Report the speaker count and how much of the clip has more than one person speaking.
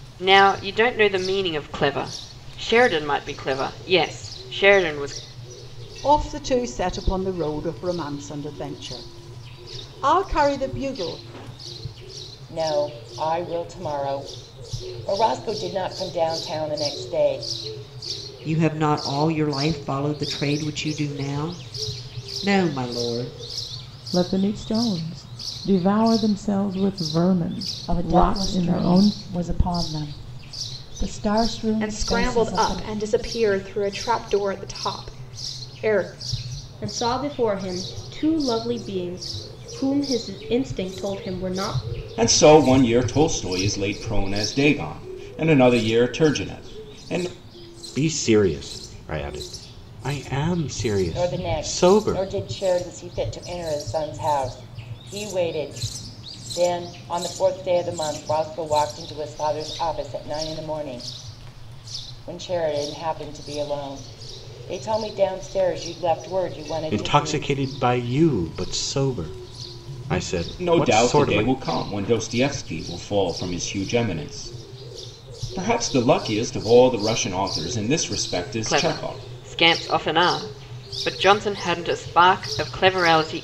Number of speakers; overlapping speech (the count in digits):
10, about 7%